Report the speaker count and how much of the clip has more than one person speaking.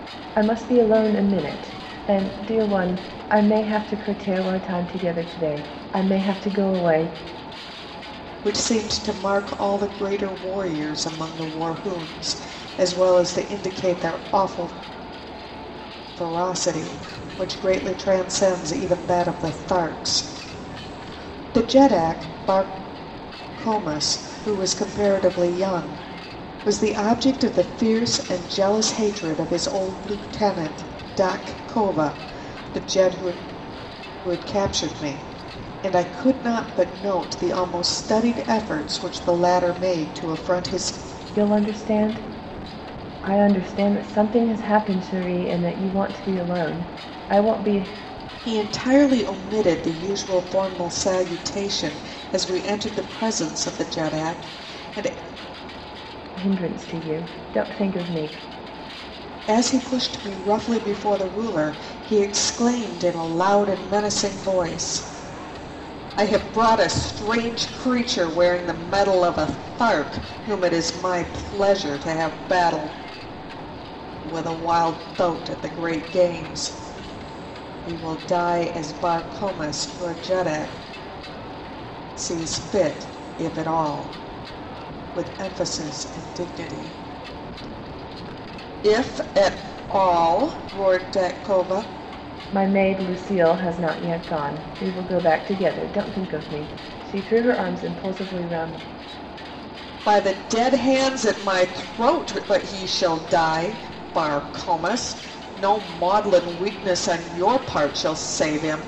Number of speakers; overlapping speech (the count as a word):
two, no overlap